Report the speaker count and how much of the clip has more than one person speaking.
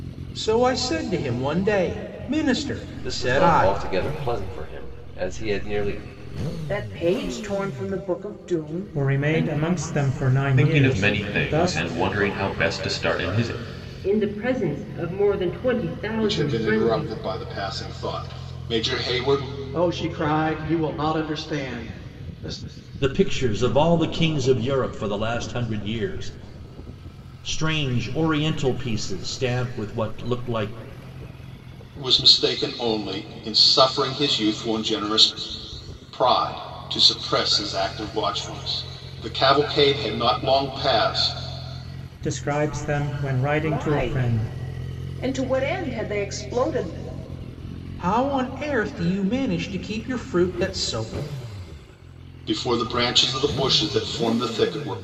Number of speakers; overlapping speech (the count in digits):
9, about 9%